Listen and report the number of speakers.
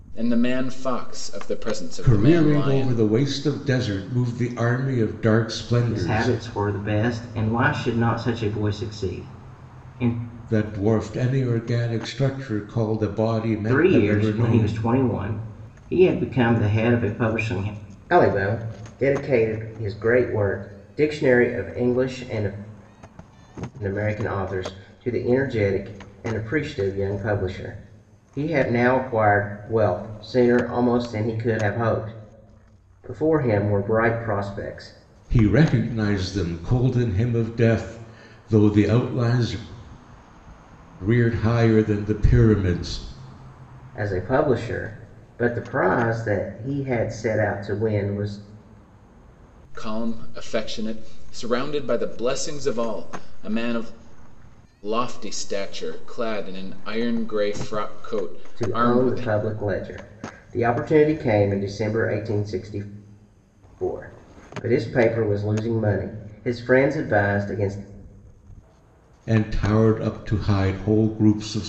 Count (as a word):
three